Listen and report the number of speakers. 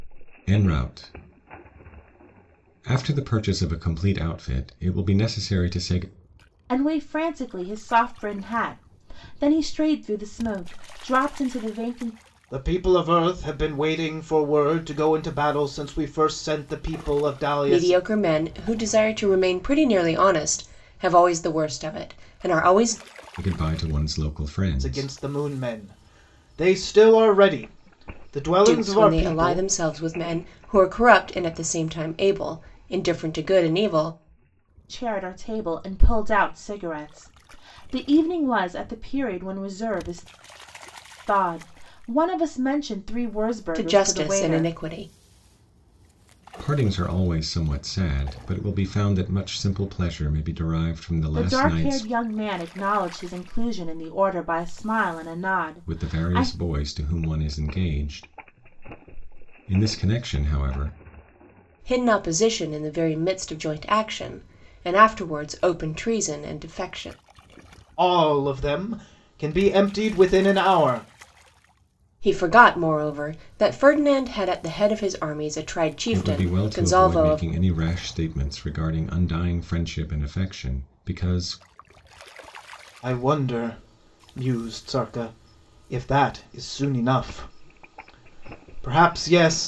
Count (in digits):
4